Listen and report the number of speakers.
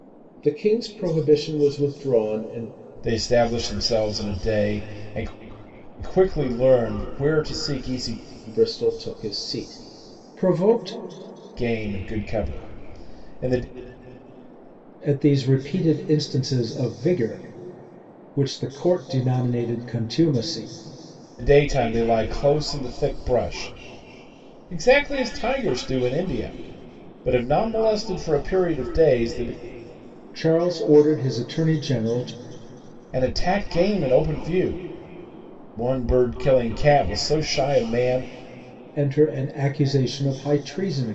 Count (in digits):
2